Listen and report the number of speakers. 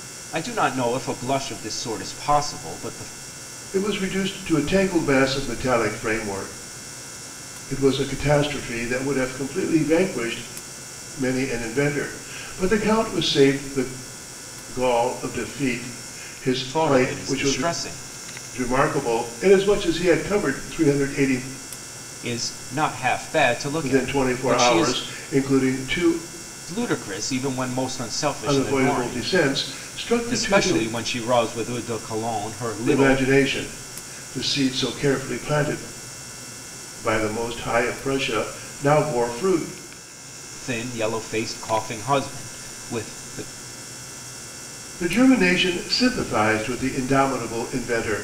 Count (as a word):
two